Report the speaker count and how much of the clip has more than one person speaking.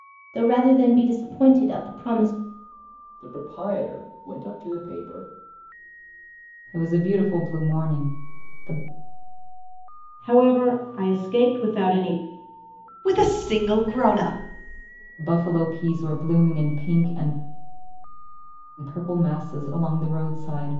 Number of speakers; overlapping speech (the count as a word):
five, no overlap